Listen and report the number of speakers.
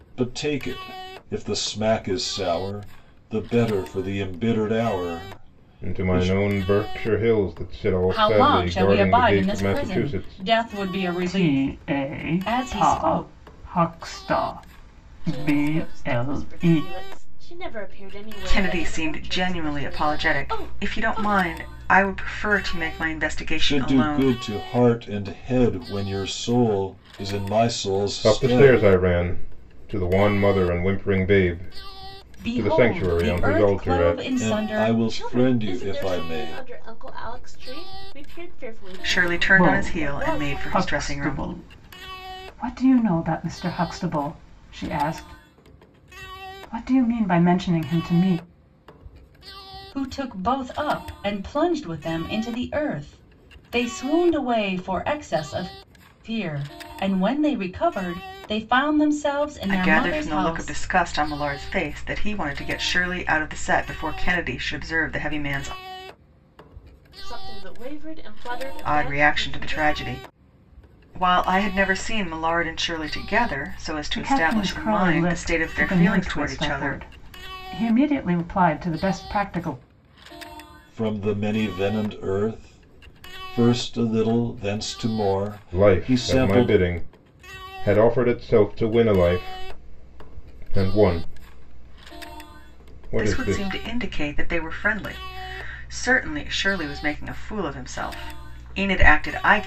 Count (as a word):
six